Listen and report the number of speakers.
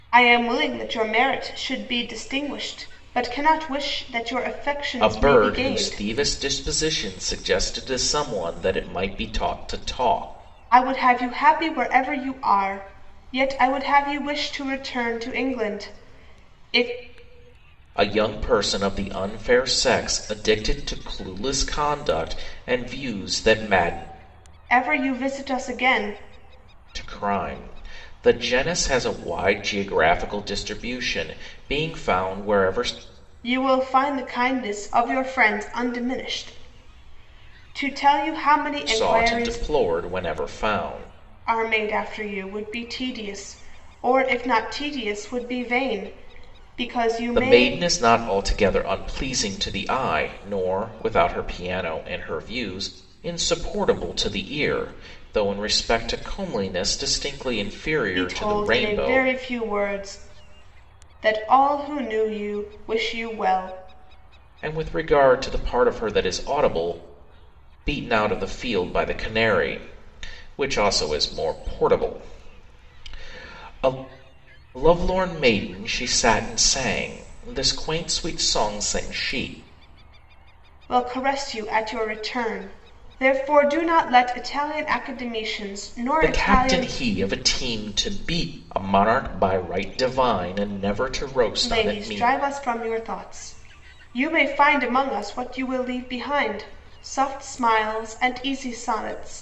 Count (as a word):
two